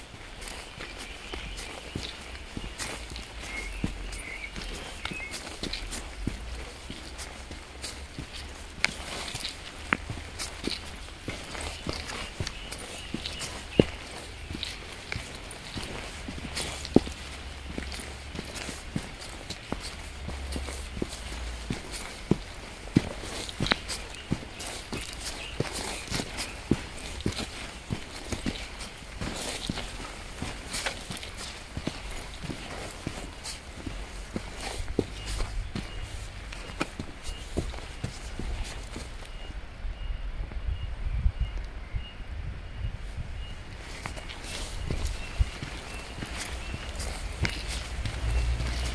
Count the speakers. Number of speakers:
zero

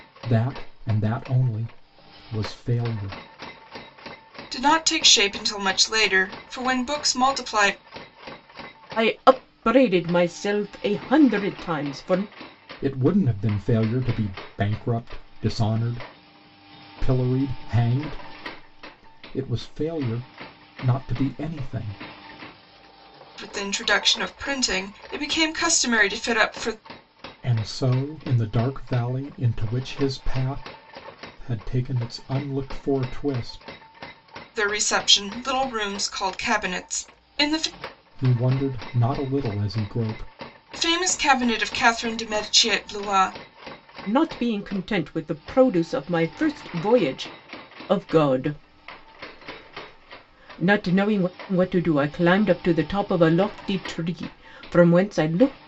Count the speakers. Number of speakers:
three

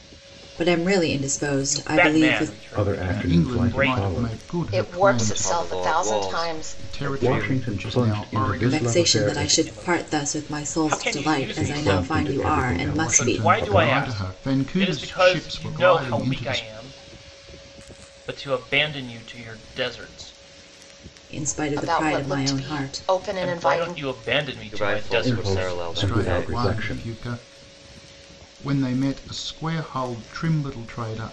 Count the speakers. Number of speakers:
six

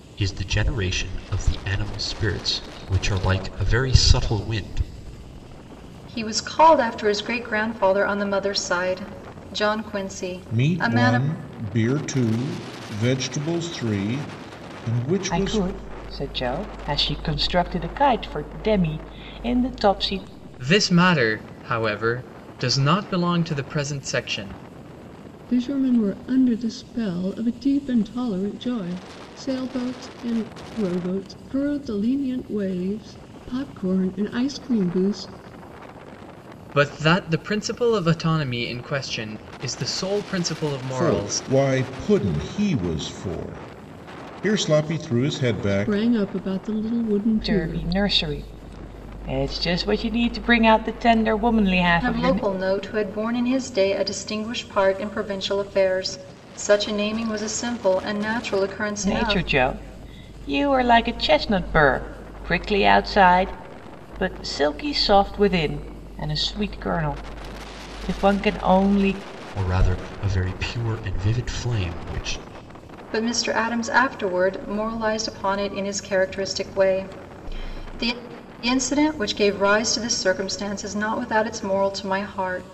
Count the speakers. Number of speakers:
six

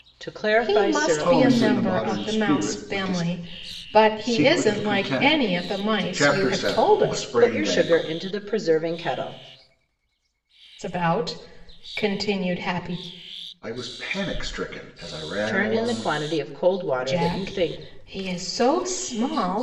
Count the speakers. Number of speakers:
three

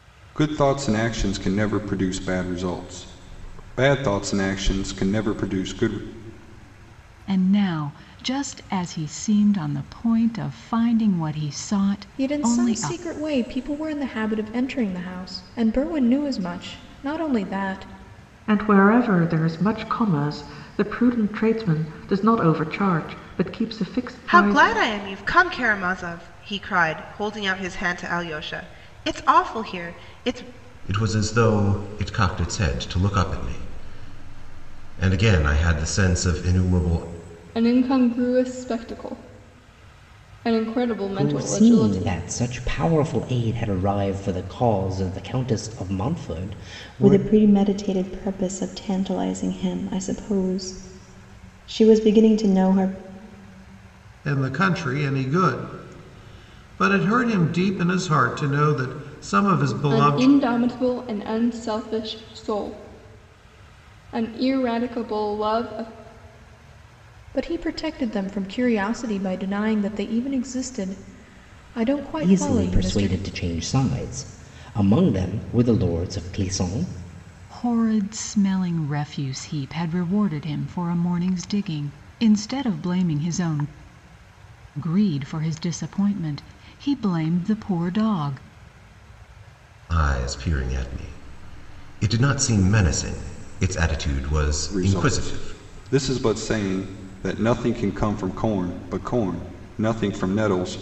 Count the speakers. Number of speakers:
ten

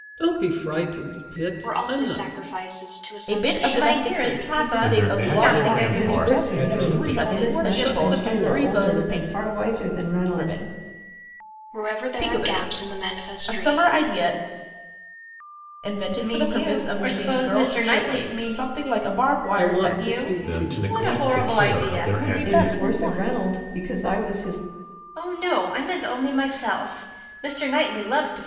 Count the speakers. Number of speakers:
seven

